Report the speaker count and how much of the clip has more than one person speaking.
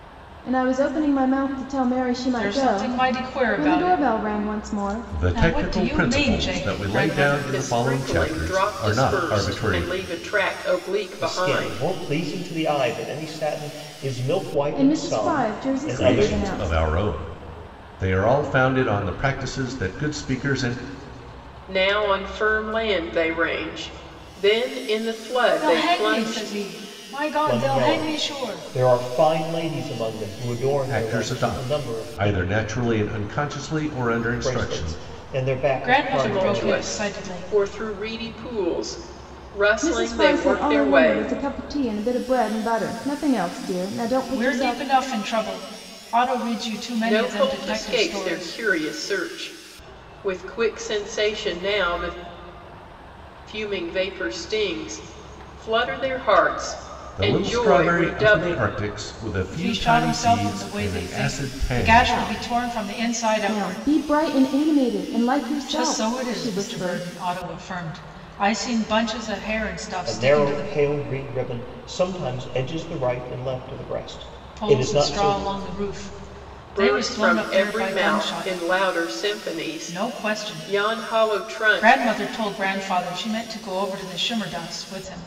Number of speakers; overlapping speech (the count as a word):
five, about 39%